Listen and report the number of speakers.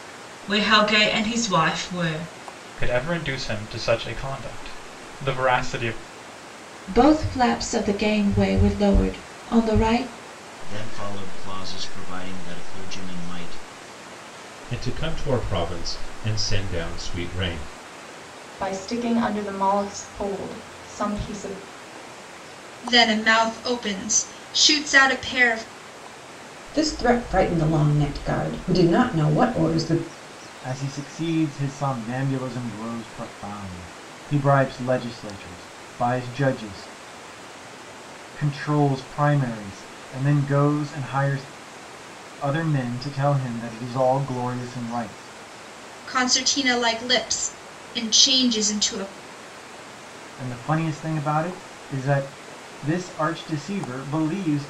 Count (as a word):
nine